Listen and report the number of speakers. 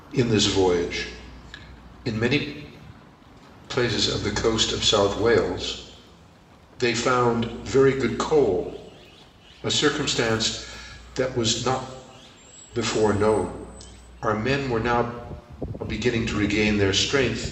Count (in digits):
1